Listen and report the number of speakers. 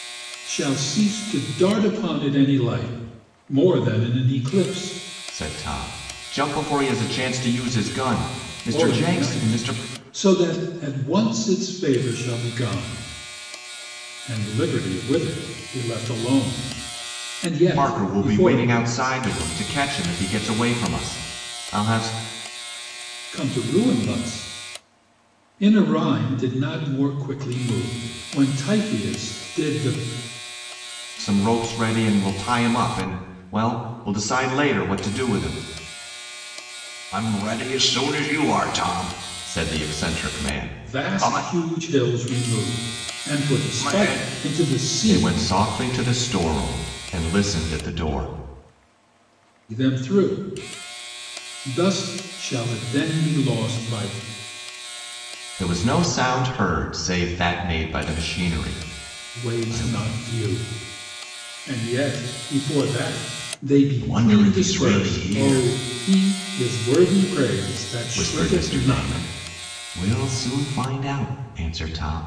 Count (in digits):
2